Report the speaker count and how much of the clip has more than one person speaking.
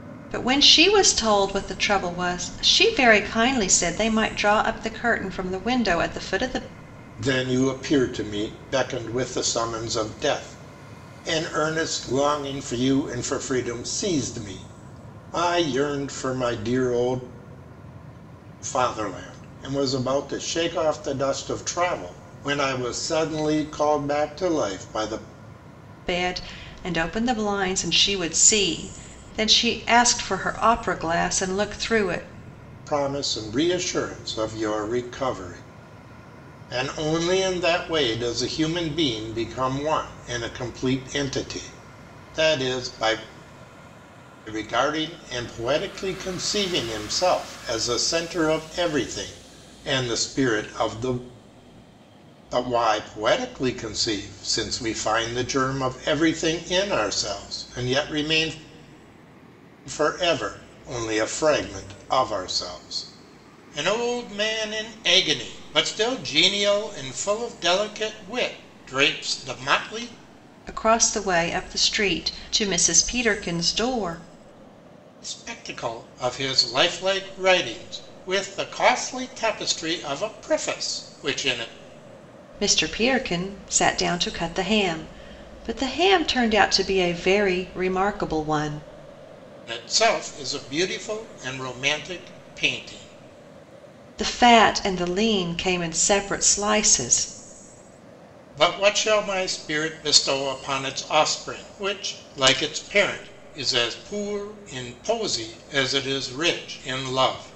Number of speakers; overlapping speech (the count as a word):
two, no overlap